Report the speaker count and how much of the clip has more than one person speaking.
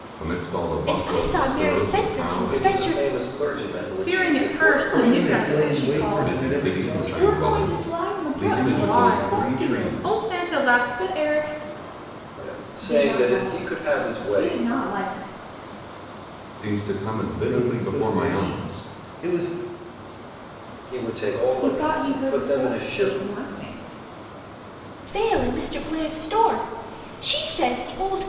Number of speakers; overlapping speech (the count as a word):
six, about 48%